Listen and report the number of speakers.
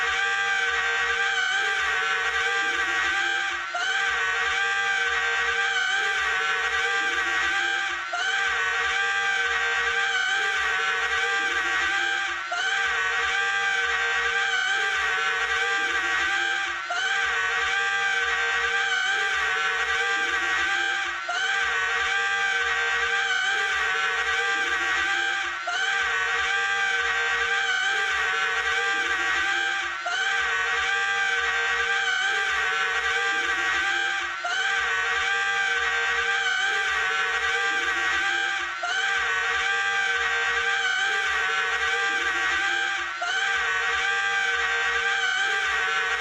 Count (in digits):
0